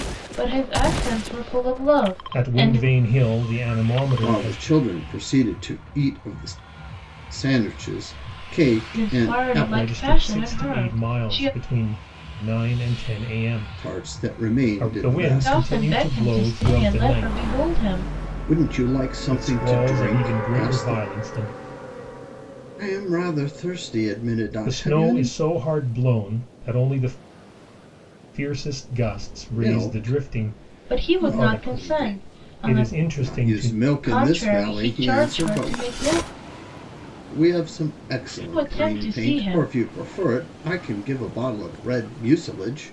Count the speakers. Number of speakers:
3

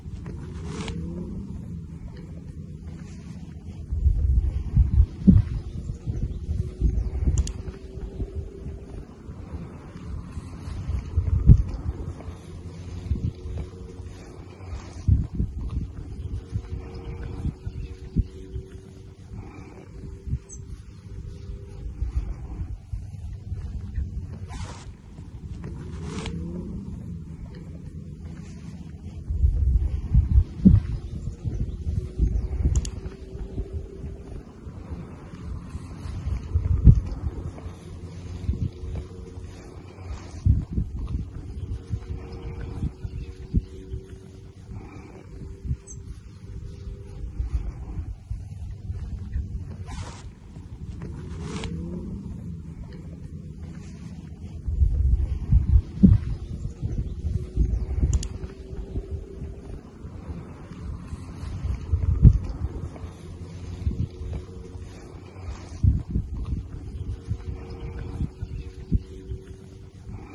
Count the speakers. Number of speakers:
0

